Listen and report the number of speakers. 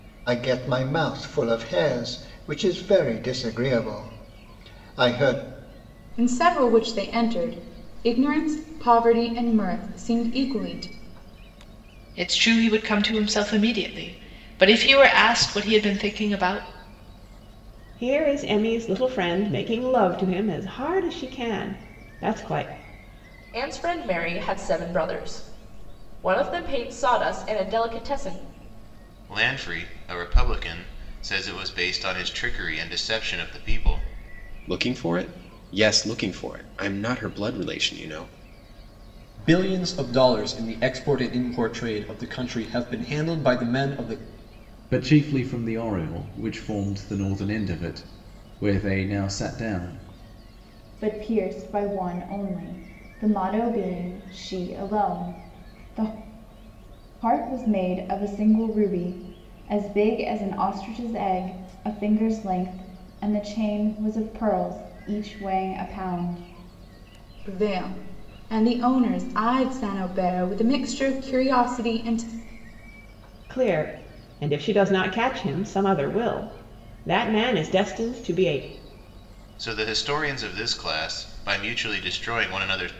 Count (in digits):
10